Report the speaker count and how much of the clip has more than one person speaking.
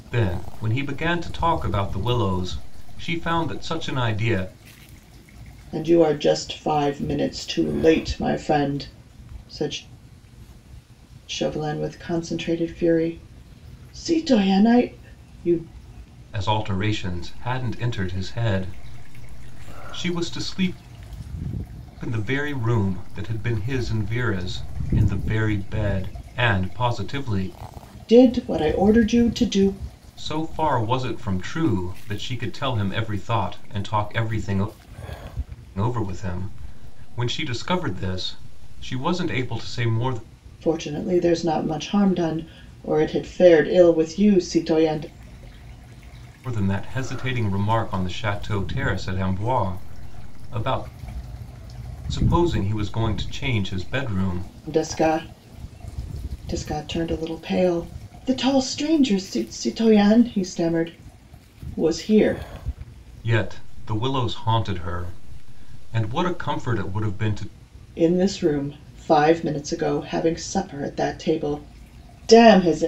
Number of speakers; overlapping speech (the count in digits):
2, no overlap